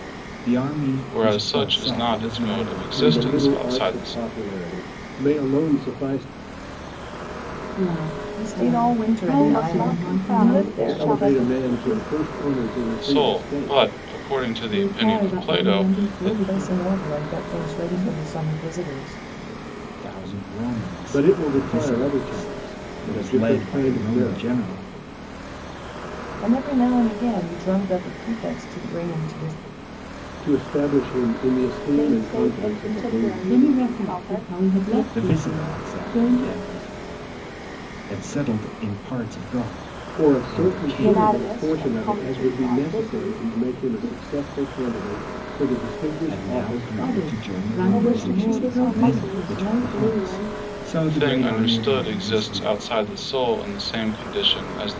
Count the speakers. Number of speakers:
six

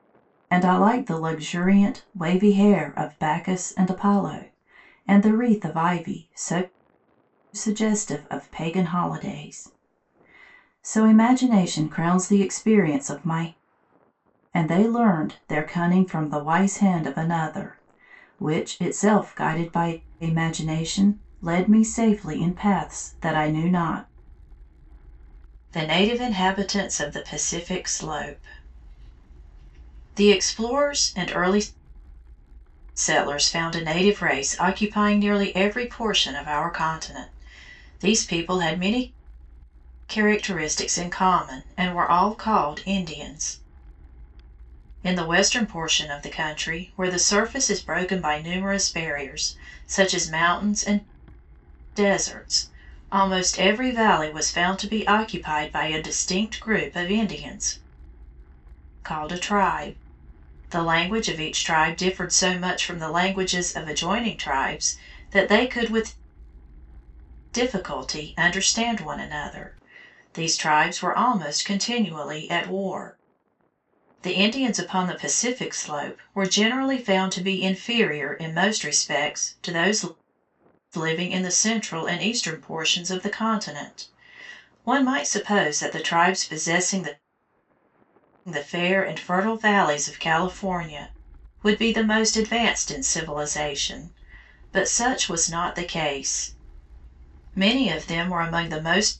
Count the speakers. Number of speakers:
one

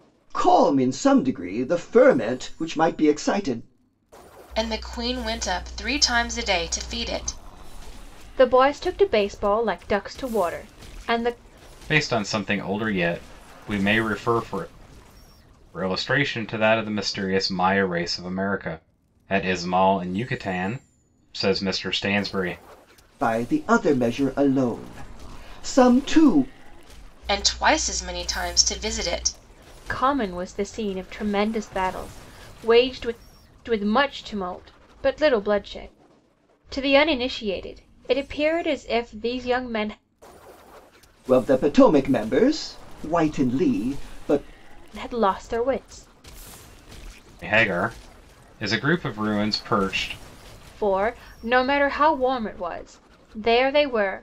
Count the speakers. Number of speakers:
four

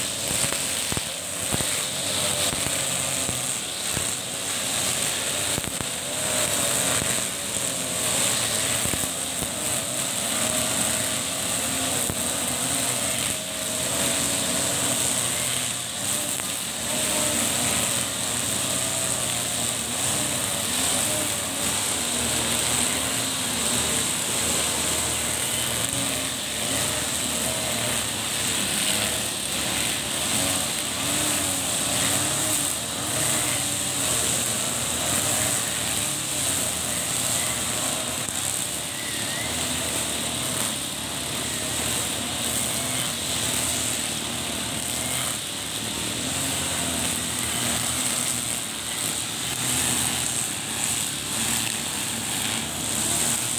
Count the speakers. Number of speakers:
zero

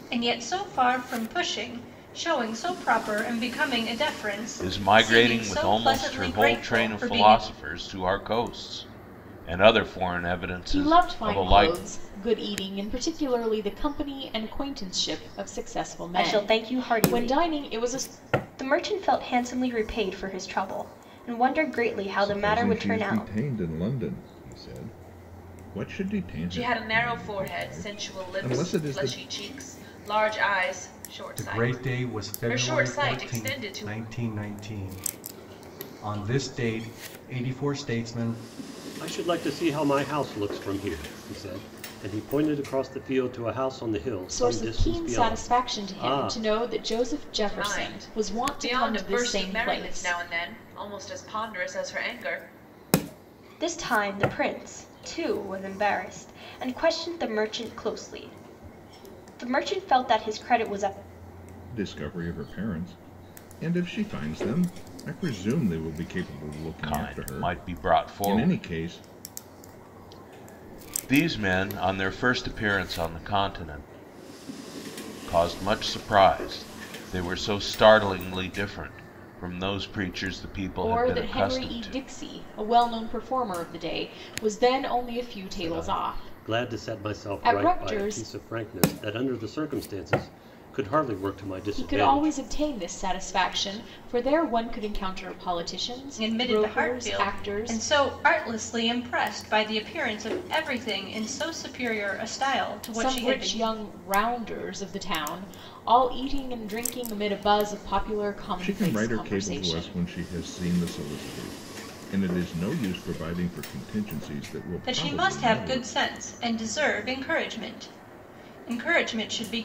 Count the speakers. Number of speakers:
eight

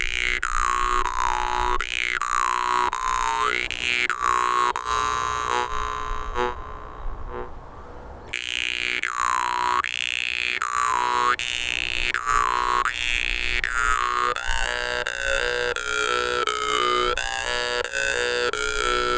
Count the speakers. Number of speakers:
zero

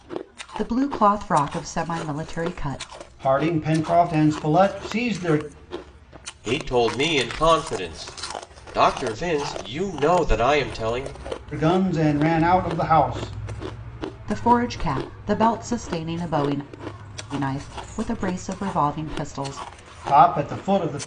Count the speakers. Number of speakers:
three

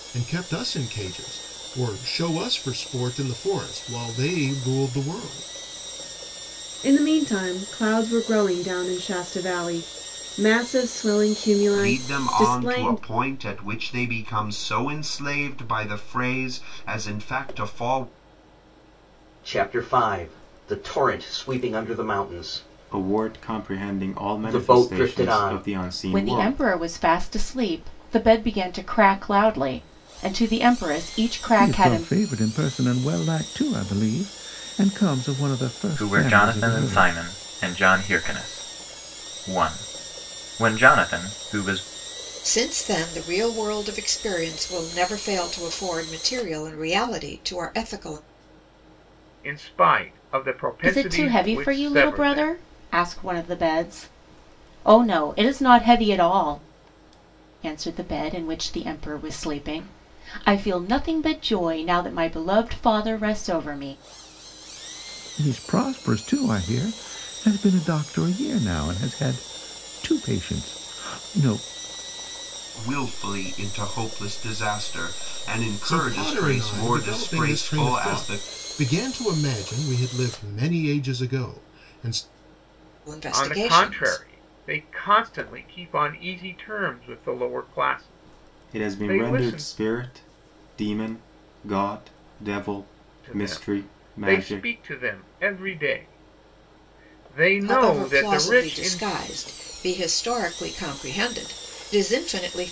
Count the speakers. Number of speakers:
ten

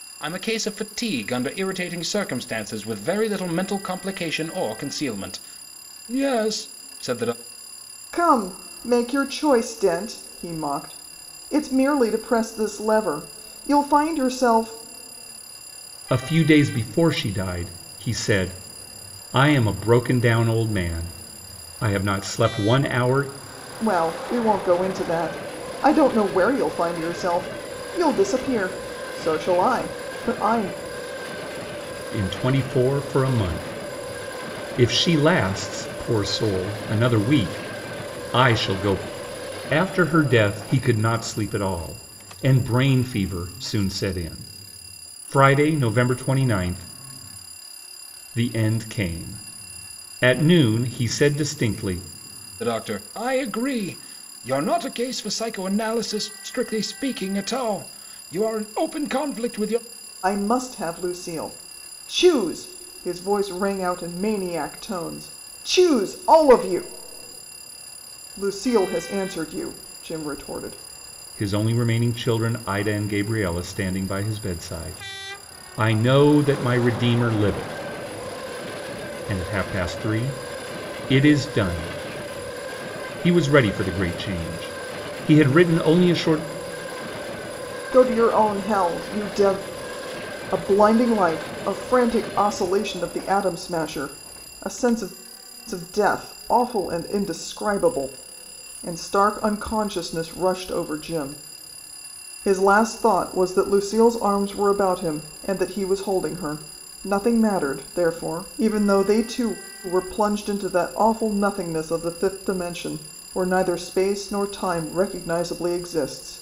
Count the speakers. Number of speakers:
three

